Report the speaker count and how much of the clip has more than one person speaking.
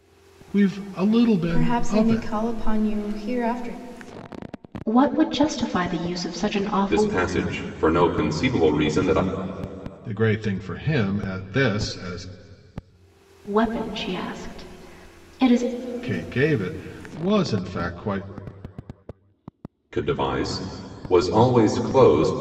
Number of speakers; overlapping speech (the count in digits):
4, about 6%